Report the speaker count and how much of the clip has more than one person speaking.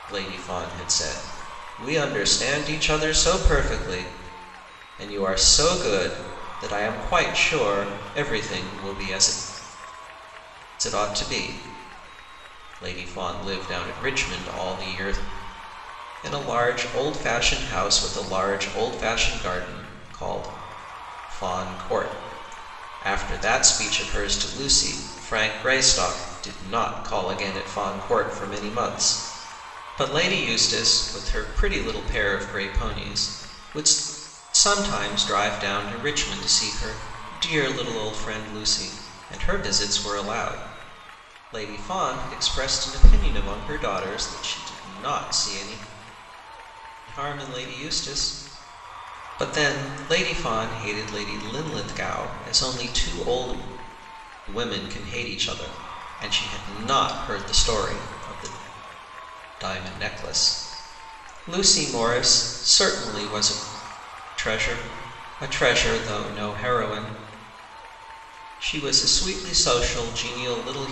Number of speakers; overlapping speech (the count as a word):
one, no overlap